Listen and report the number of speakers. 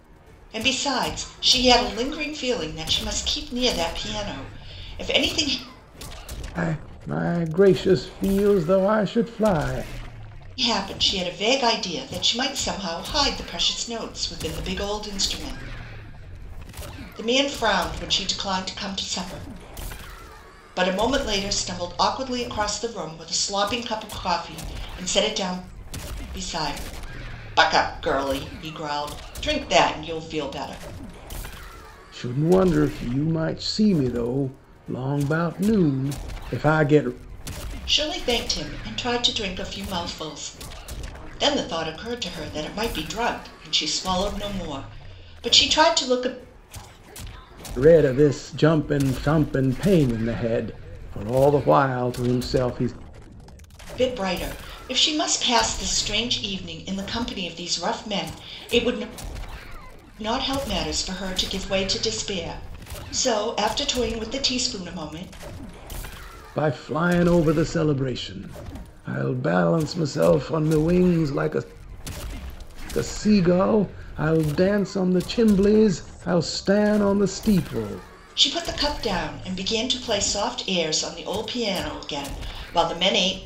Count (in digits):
2